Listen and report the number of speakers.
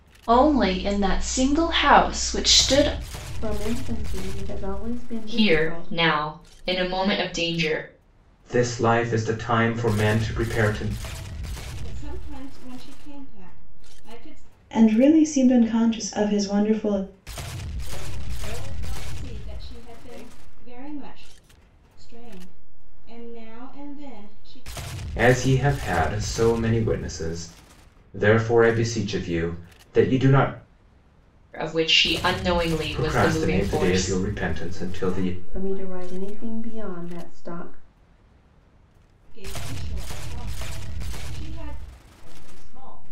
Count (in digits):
7